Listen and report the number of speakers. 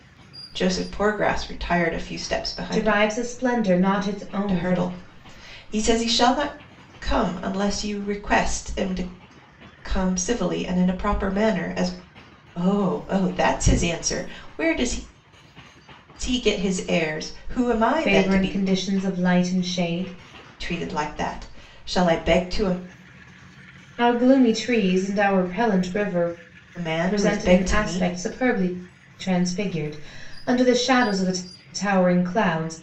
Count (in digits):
2